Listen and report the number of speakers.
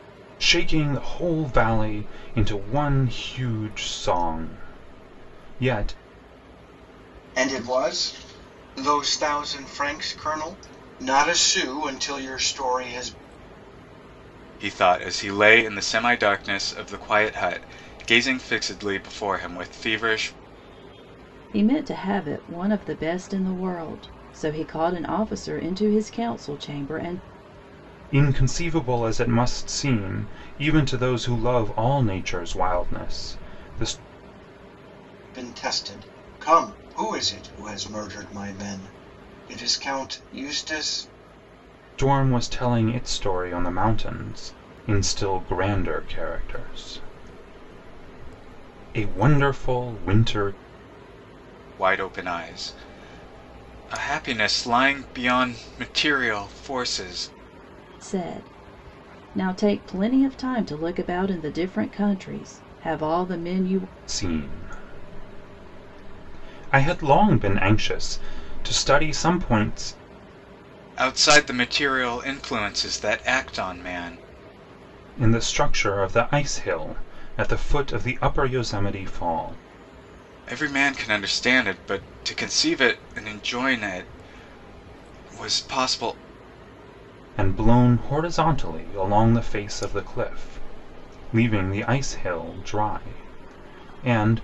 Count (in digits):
4